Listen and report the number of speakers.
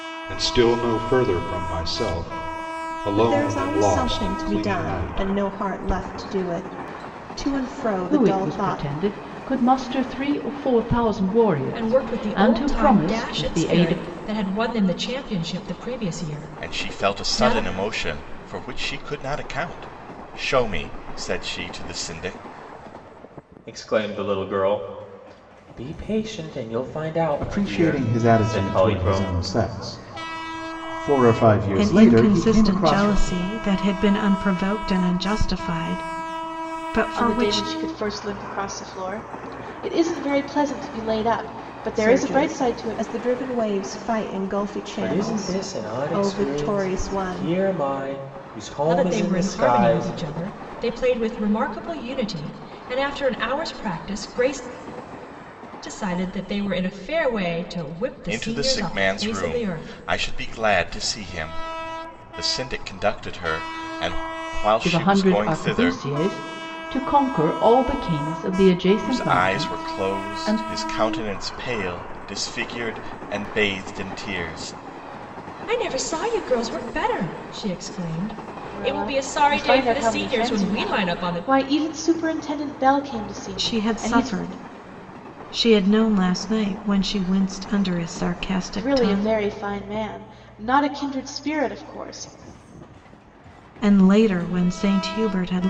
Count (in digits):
9